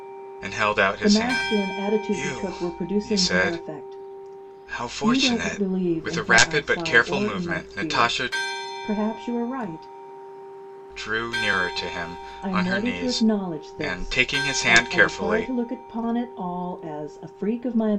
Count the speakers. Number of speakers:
2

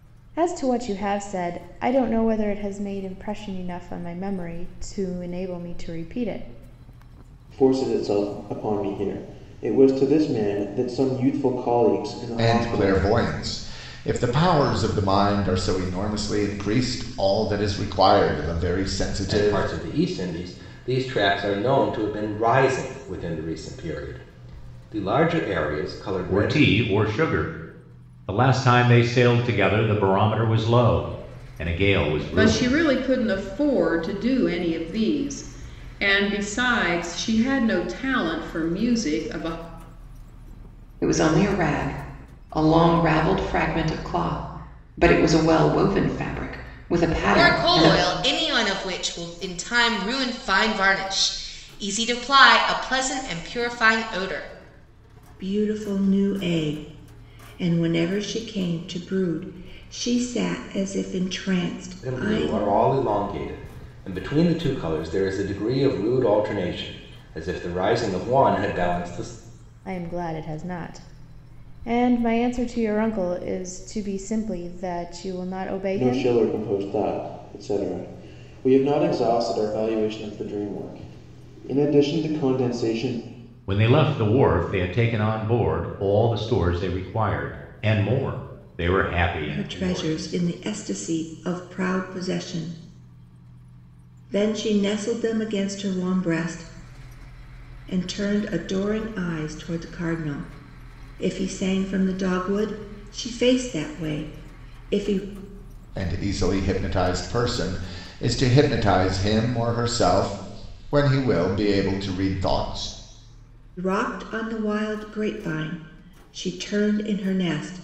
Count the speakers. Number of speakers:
9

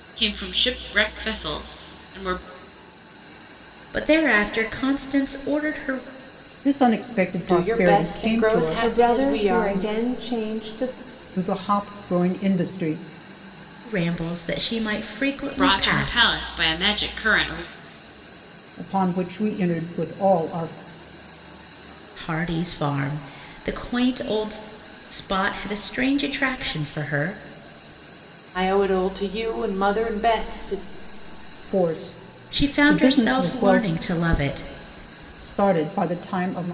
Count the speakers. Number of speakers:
5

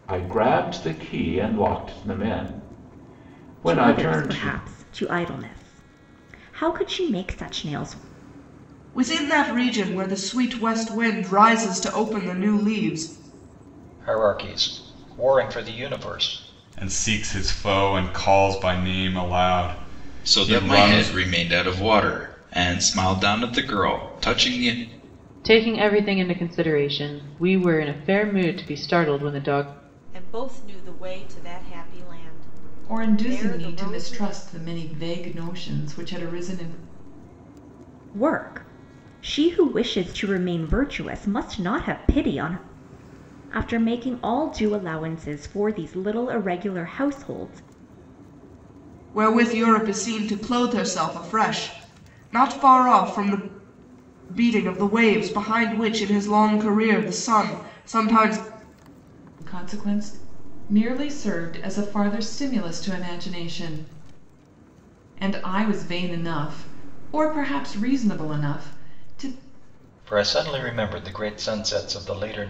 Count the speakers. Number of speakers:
9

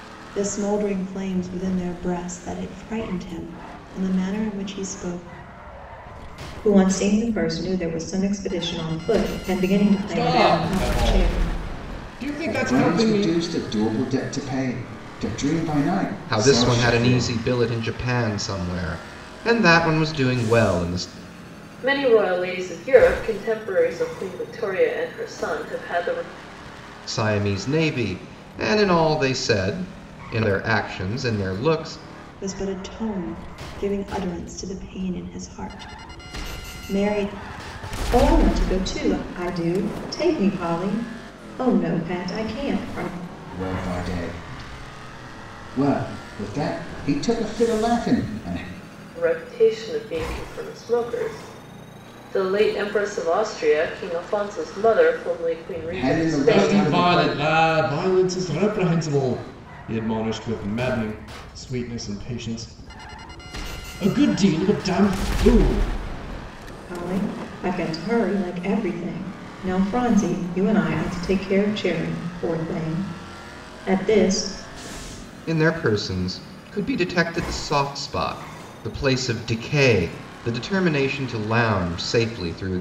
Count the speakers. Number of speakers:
6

